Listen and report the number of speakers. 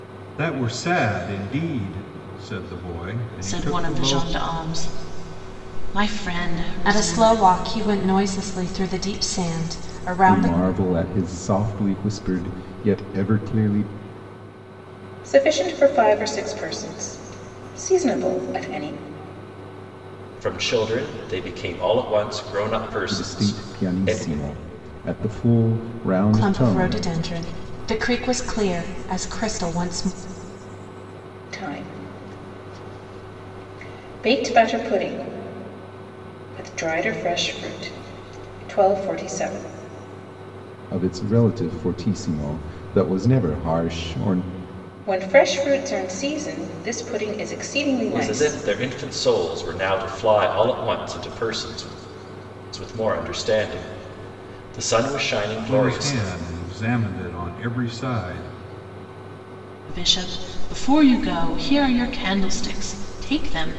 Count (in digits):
6